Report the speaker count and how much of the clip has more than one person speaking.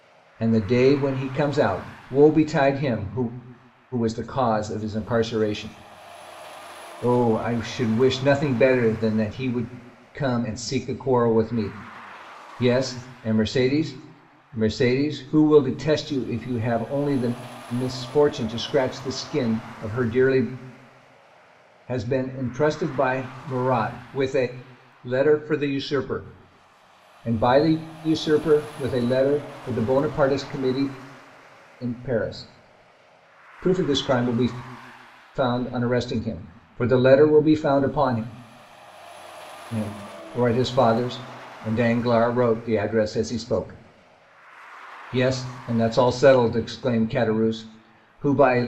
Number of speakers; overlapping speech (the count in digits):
1, no overlap